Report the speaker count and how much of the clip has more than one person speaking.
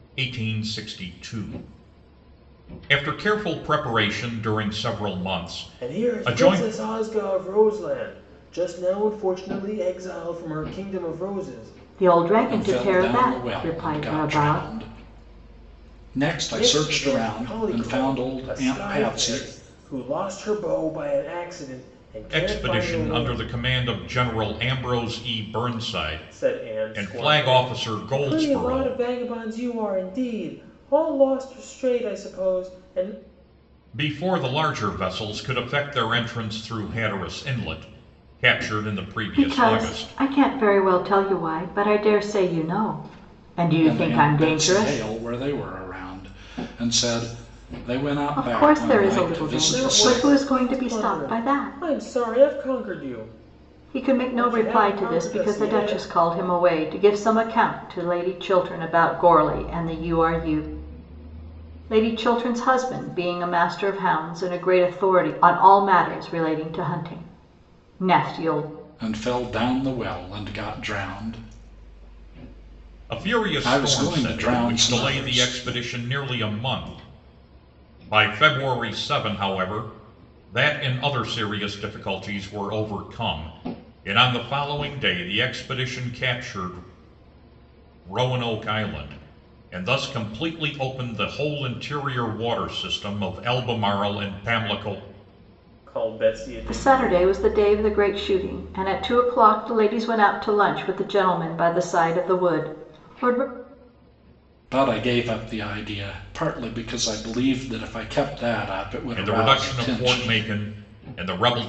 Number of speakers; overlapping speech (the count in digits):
4, about 20%